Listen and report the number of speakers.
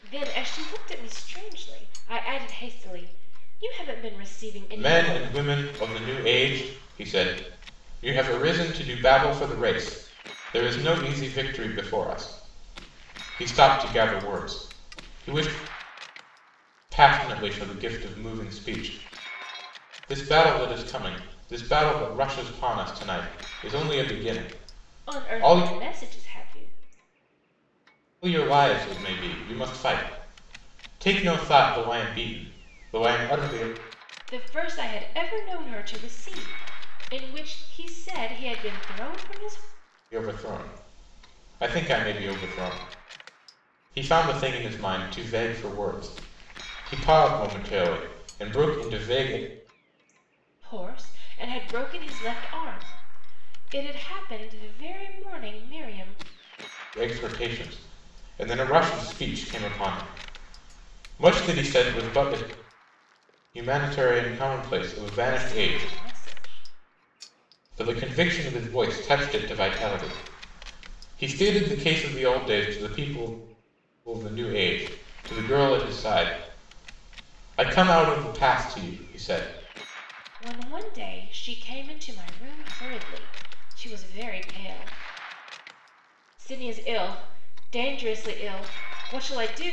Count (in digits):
2